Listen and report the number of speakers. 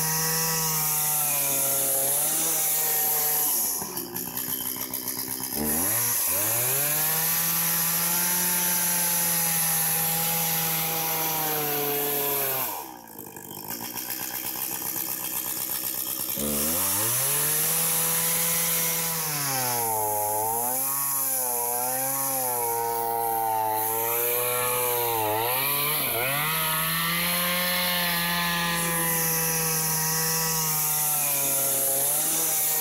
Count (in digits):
0